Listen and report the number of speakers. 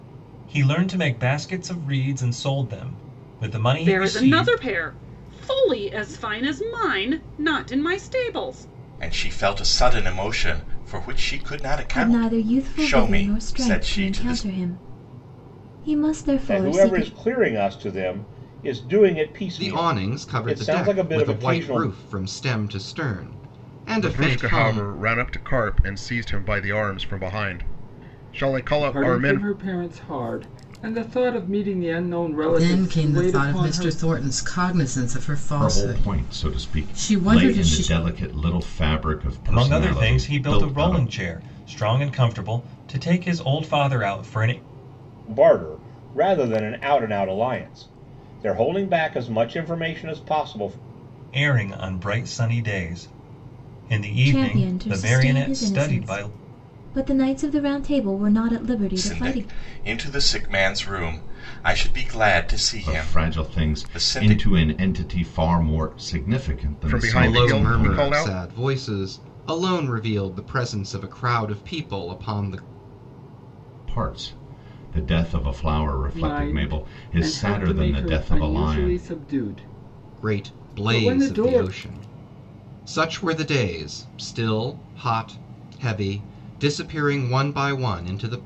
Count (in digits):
10